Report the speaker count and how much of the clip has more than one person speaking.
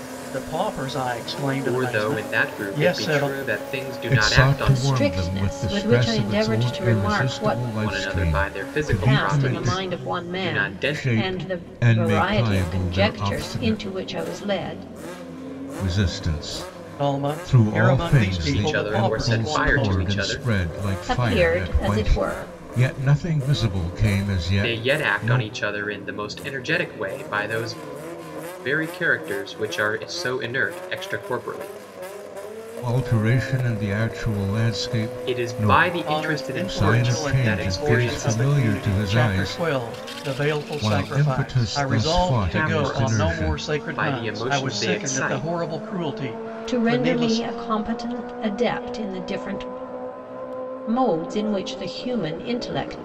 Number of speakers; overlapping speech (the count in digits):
4, about 50%